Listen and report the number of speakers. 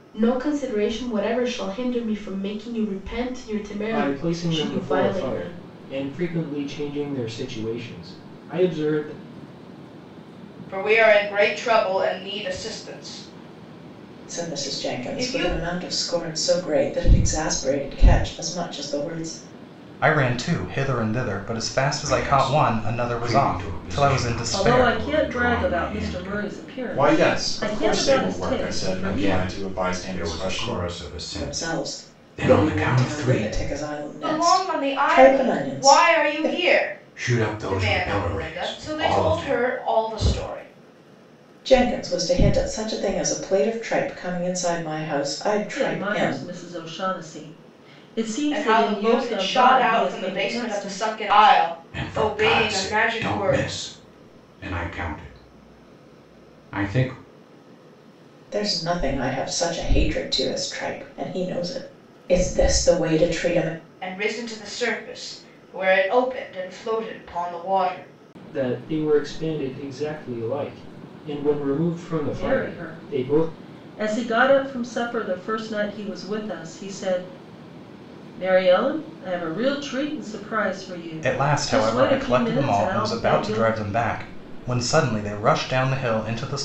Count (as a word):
eight